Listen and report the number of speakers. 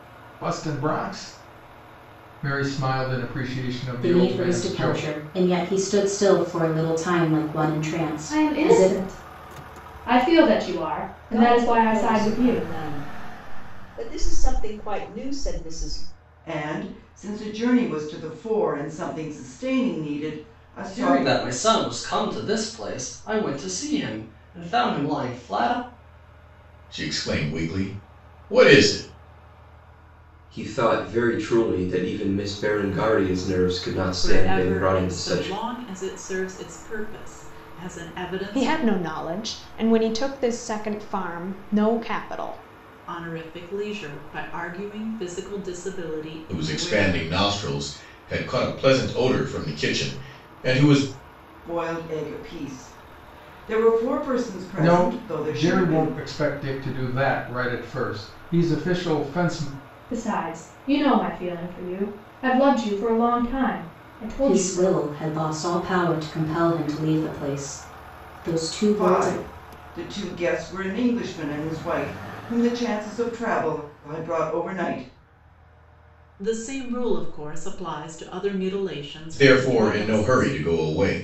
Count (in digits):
10